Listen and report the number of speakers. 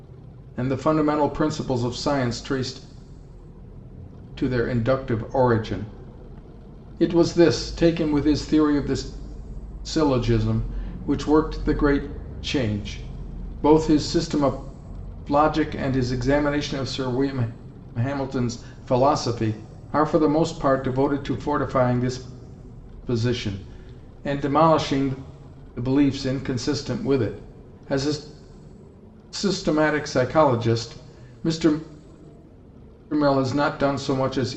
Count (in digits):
1